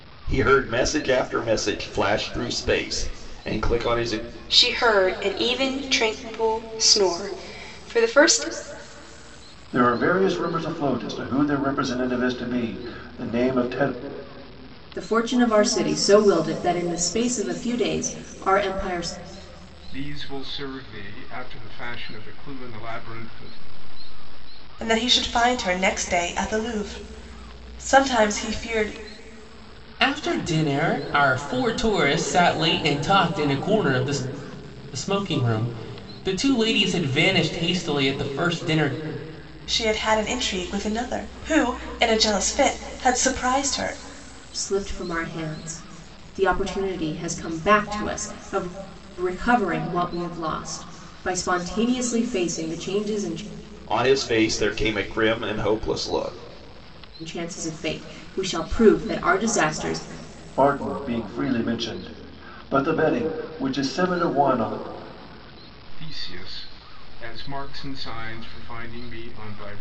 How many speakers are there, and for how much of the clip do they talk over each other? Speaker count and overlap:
7, no overlap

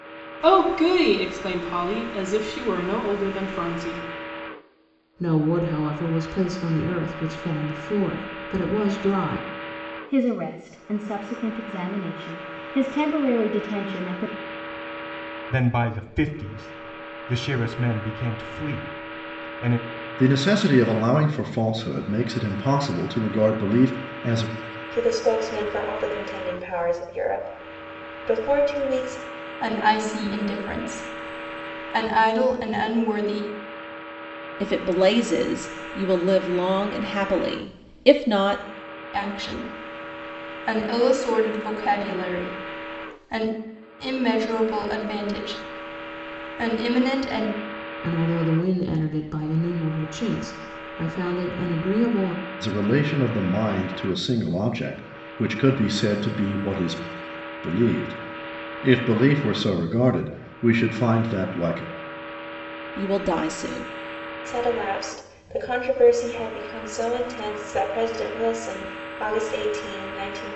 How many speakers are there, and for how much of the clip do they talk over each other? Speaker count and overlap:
8, no overlap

